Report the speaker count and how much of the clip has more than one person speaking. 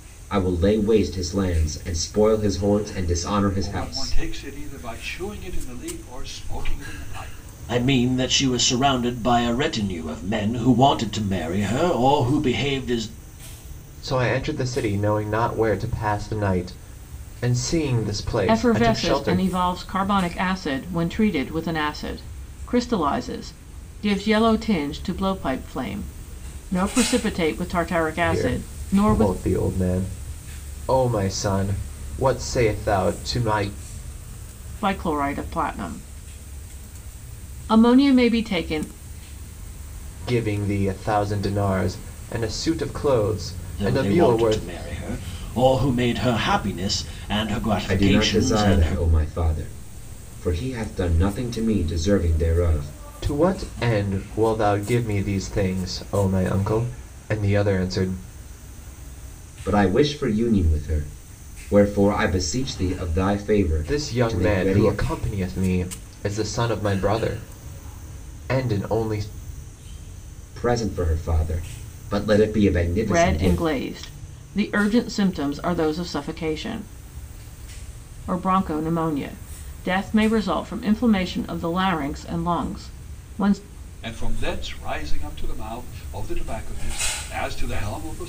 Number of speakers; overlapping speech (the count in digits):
5, about 8%